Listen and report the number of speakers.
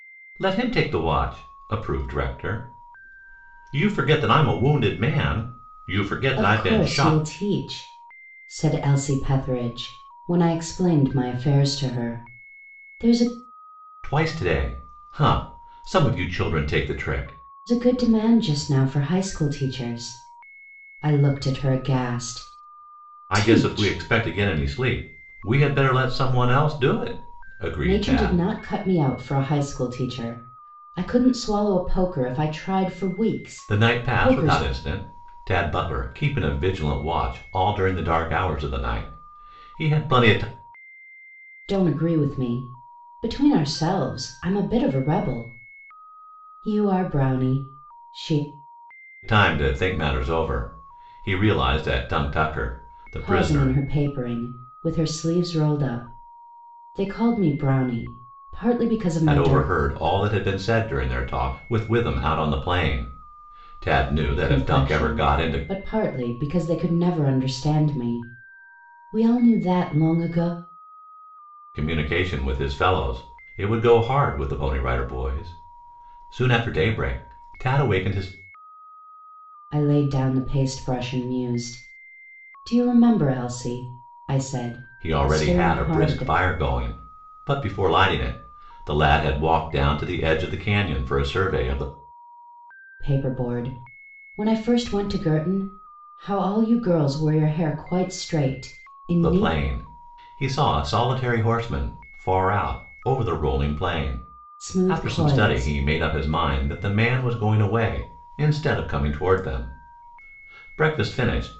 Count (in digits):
2